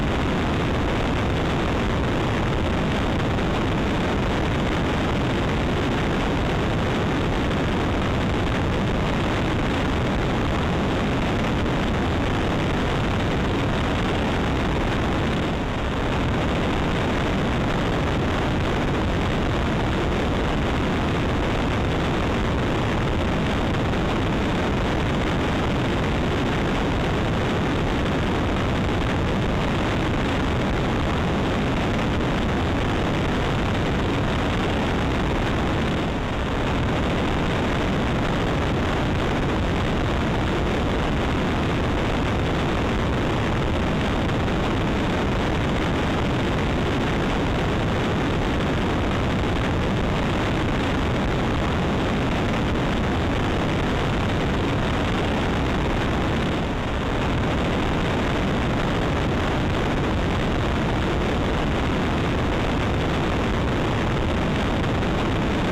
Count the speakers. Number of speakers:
0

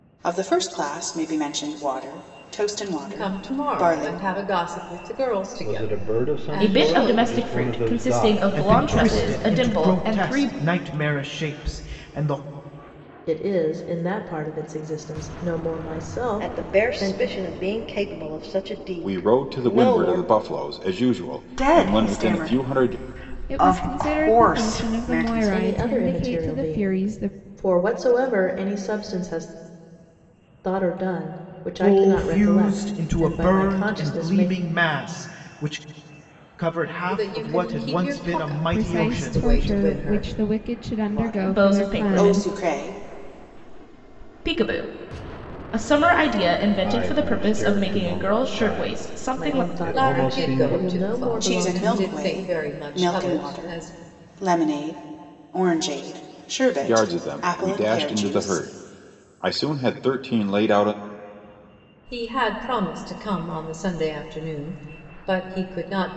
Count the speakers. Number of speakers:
10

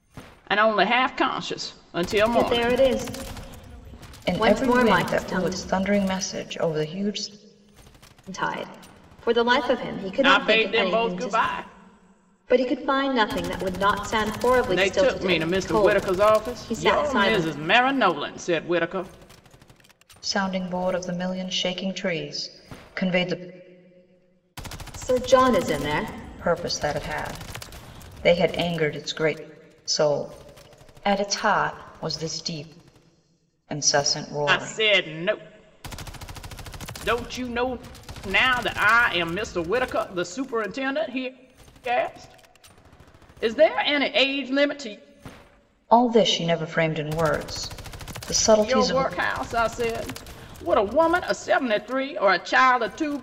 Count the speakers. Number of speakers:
3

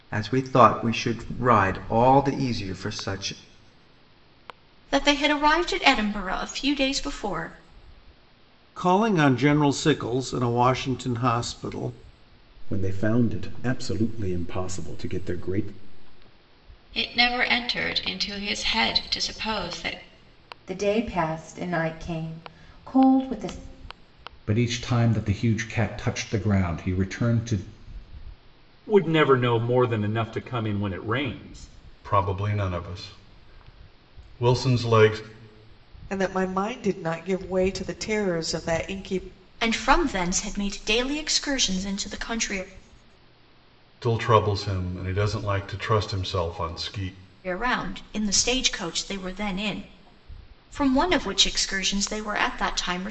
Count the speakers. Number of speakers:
10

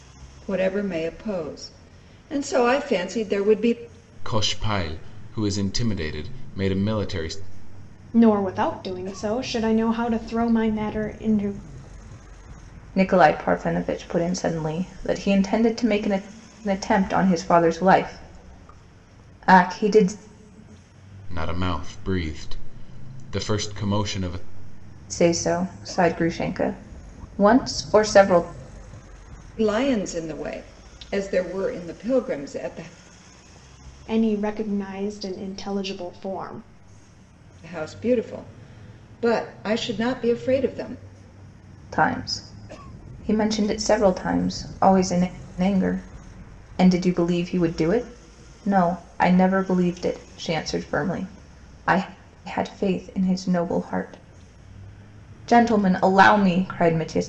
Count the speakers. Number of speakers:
4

